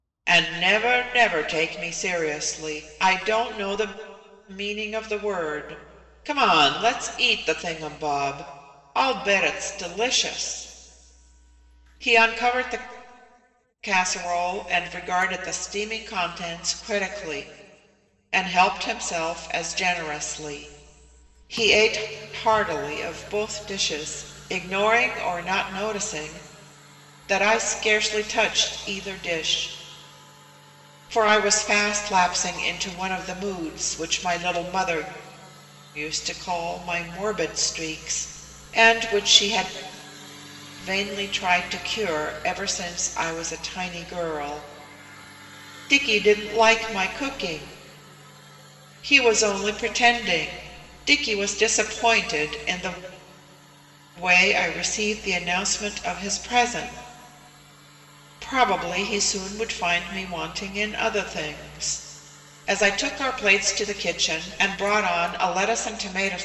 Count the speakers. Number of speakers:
1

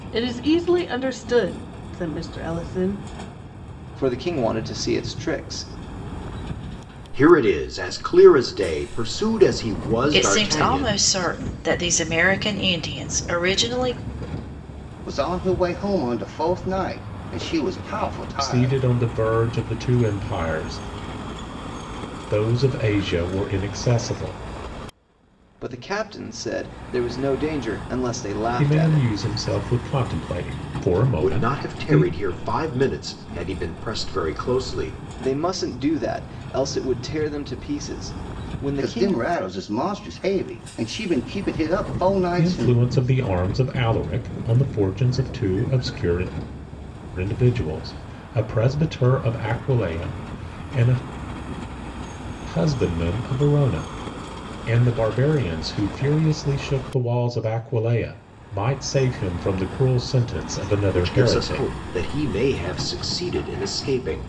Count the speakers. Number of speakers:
6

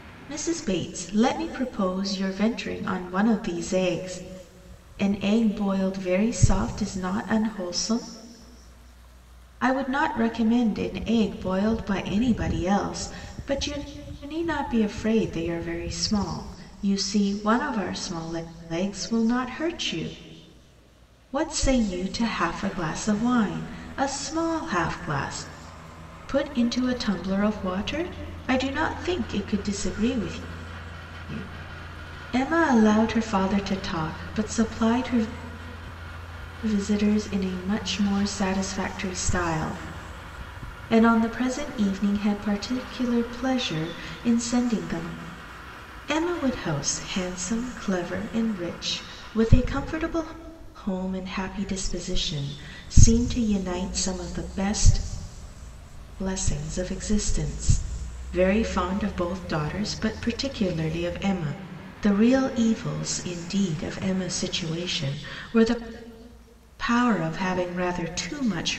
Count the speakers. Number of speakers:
1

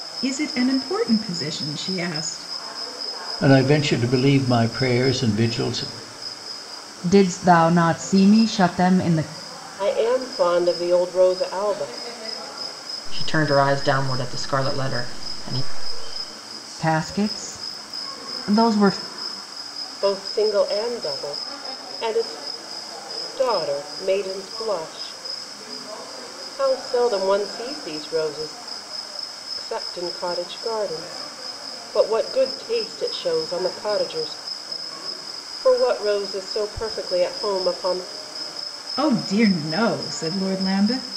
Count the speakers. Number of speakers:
5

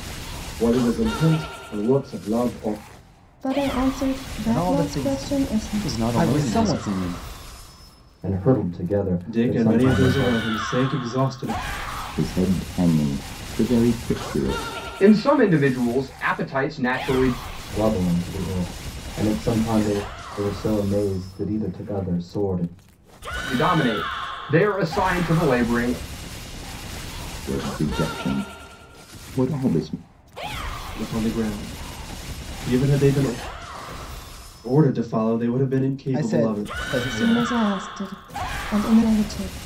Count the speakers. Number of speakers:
8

